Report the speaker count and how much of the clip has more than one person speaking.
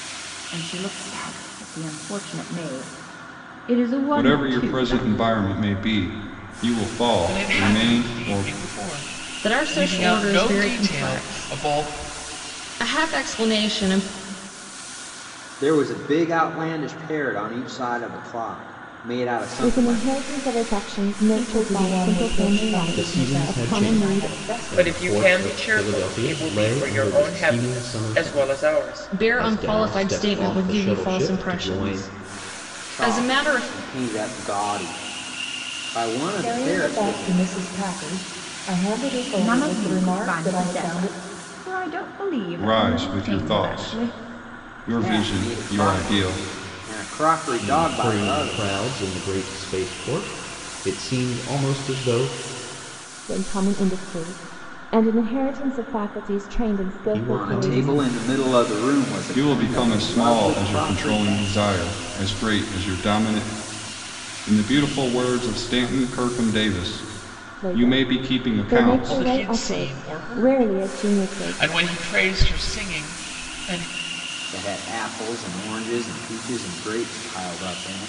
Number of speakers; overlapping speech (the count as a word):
nine, about 41%